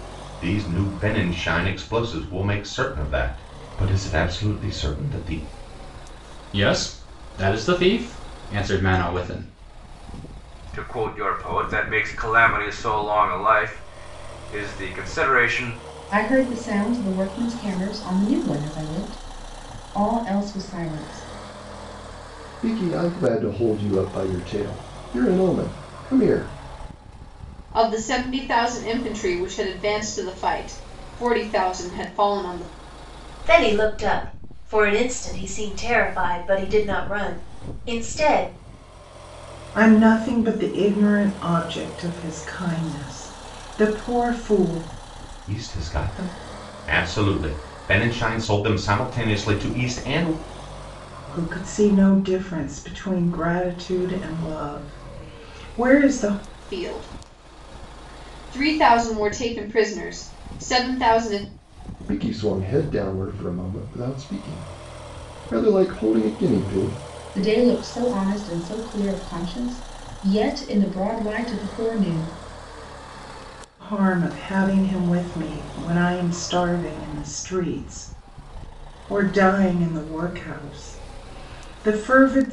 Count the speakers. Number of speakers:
eight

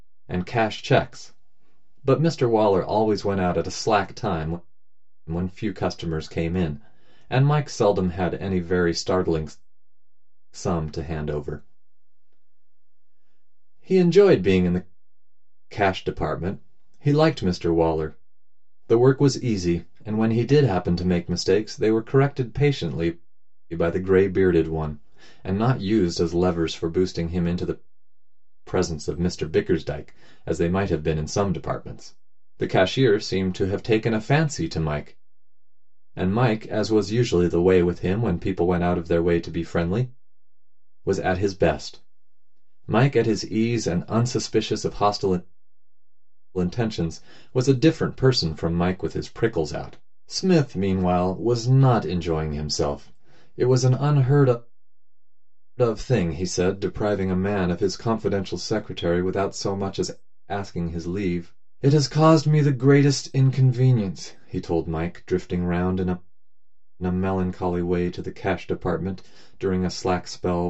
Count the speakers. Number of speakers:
one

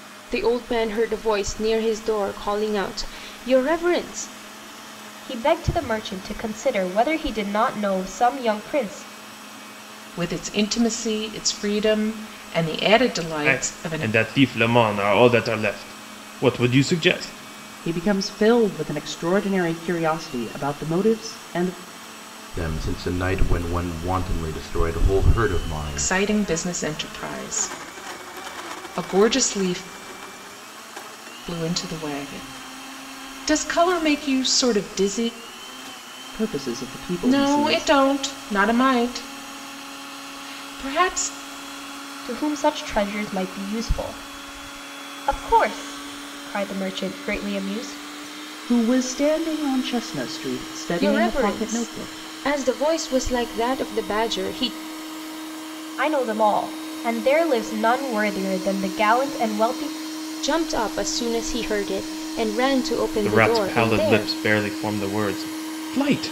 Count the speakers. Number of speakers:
six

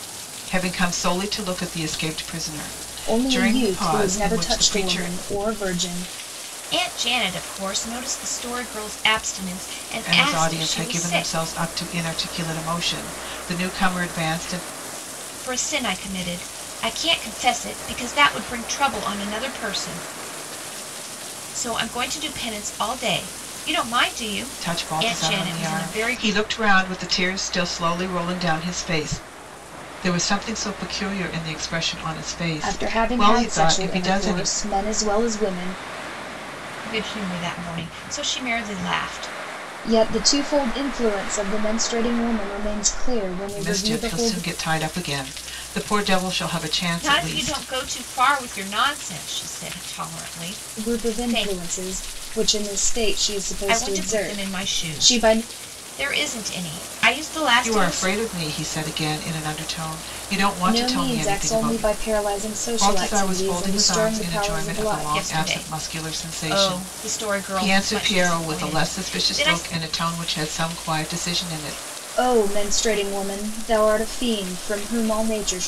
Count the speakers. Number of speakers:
three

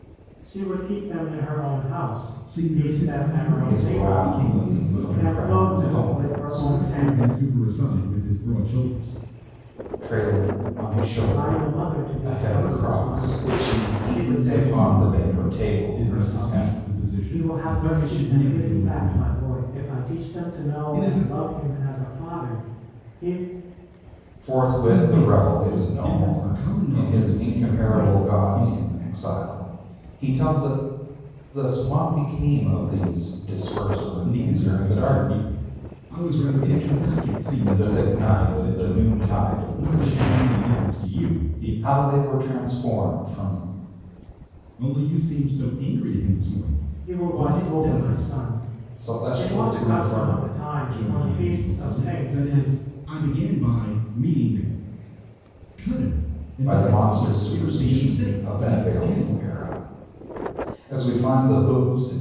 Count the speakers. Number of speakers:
three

